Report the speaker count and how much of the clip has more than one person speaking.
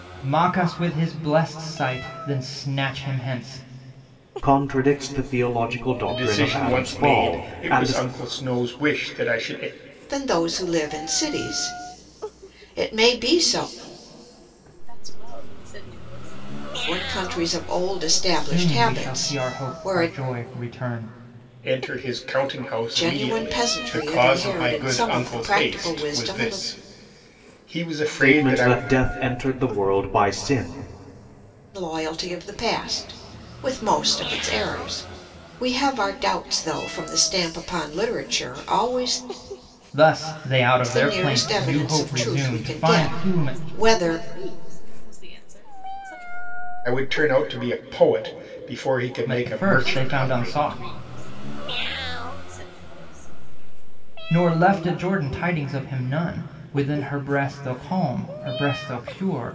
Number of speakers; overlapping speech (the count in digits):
5, about 24%